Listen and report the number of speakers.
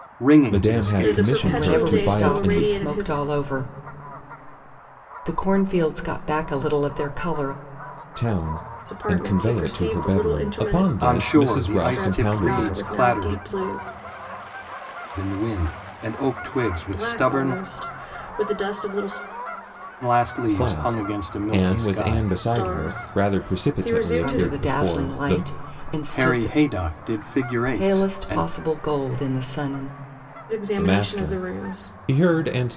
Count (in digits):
4